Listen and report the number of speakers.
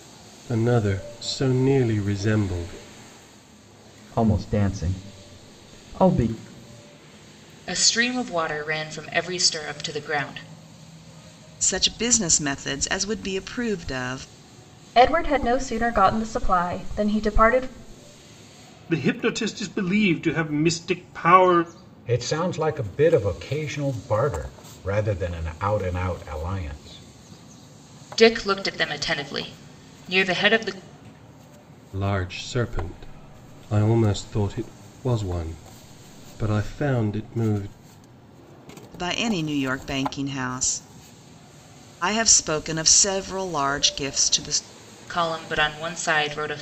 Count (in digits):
7